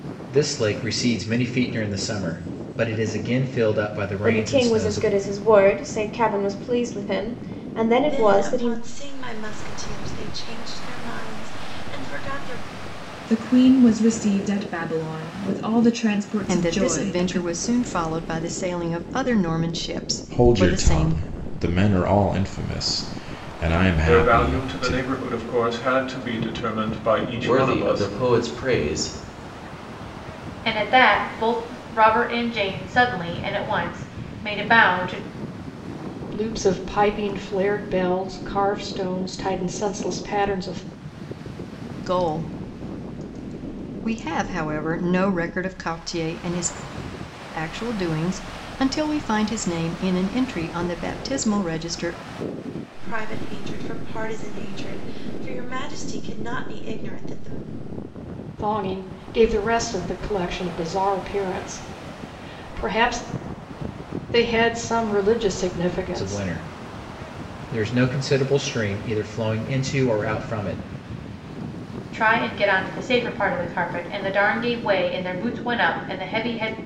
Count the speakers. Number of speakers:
10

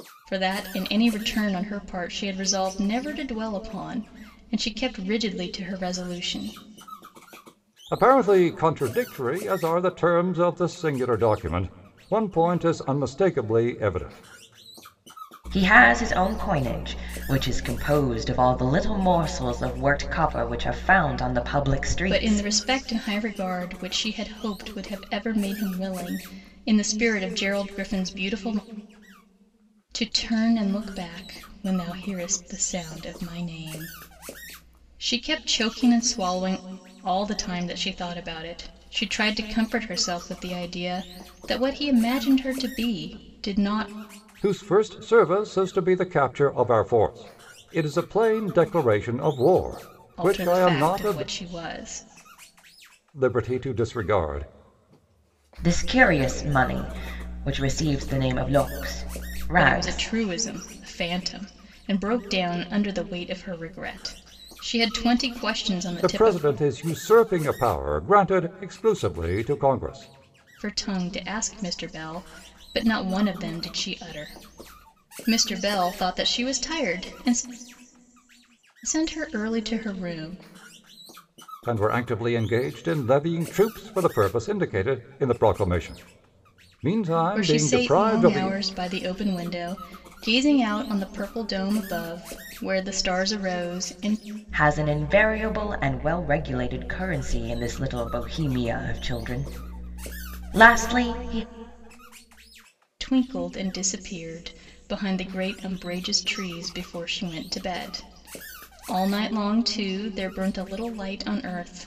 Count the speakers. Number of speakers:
3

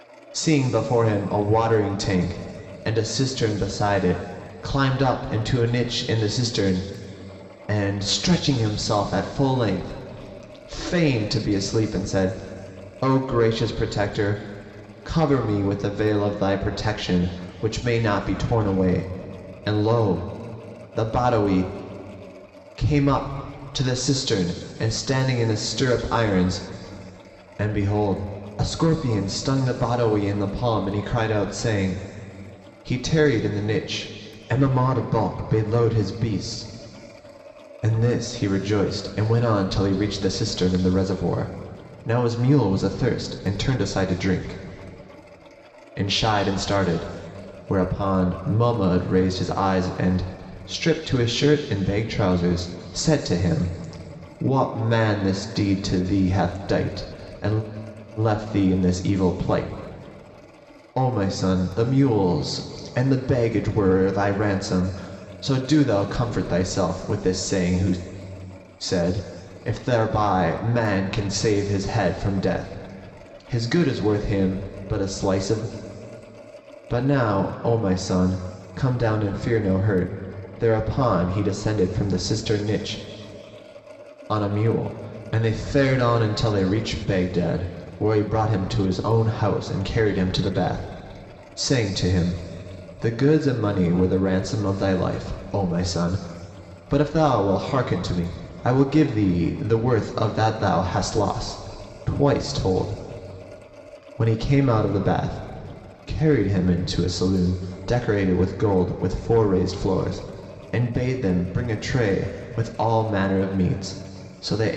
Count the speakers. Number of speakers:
1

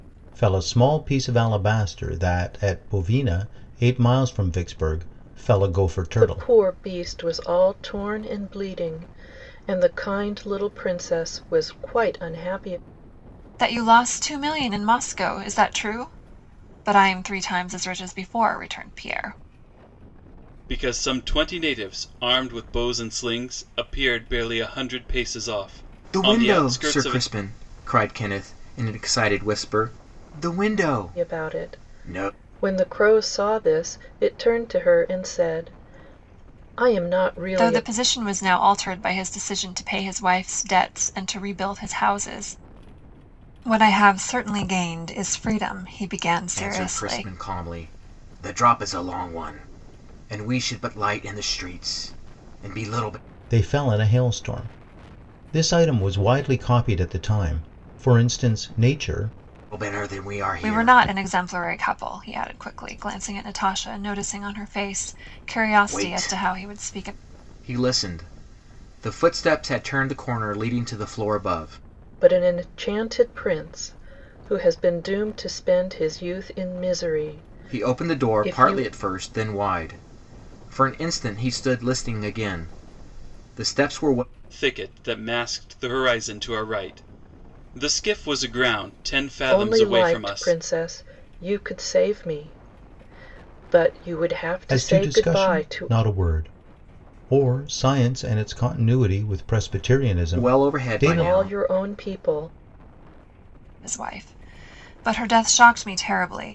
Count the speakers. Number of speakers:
5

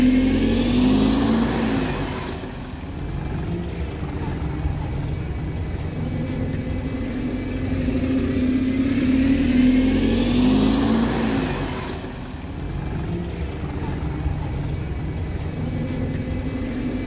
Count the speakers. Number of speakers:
0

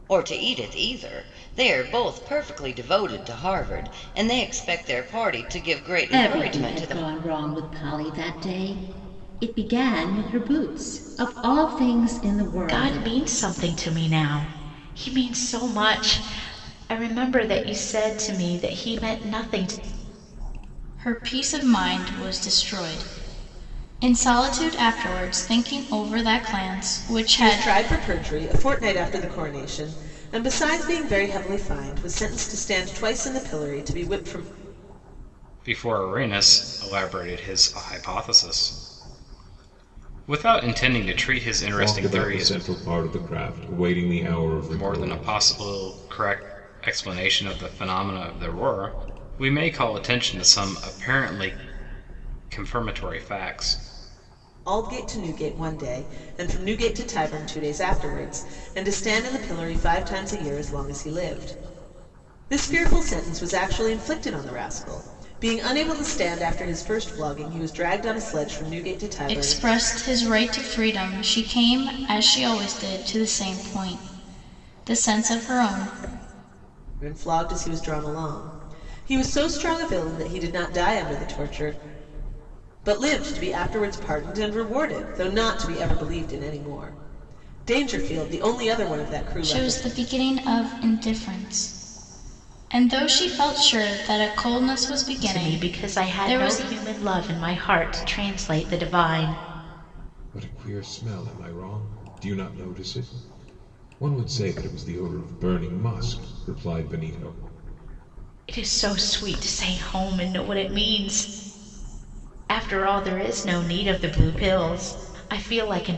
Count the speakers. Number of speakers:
7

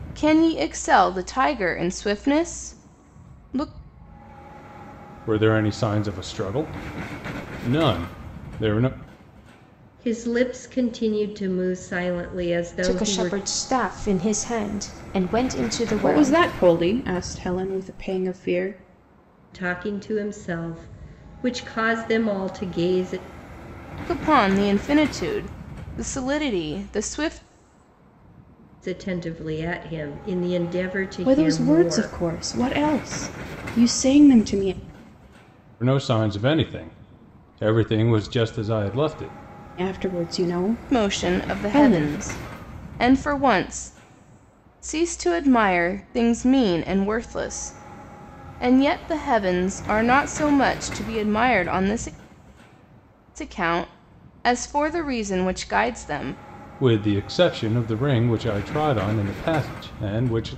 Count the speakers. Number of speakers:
5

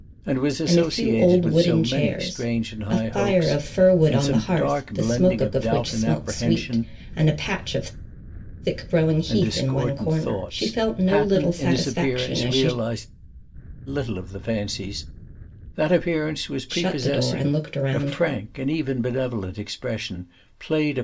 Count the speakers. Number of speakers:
2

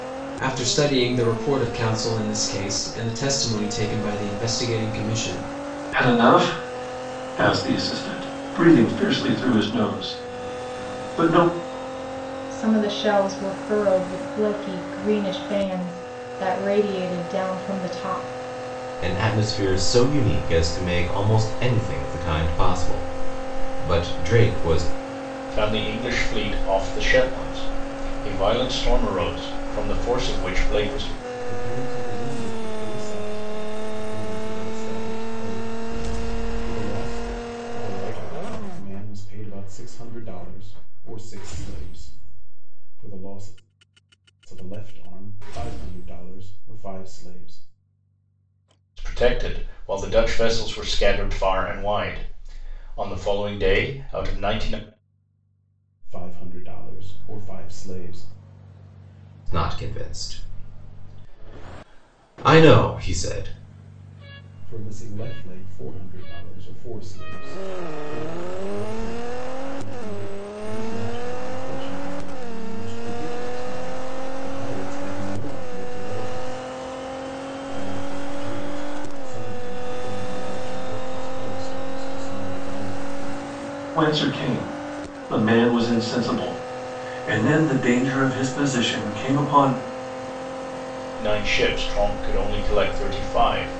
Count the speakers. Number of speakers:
6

